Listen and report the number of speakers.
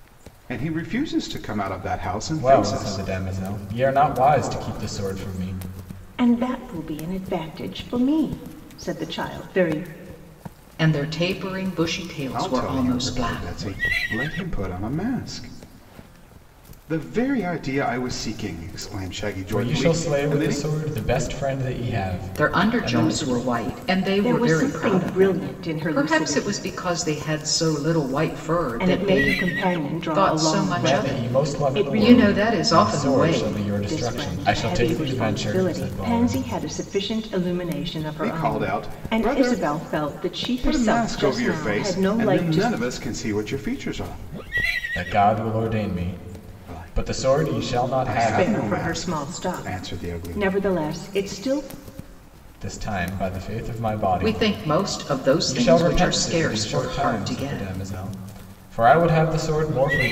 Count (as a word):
four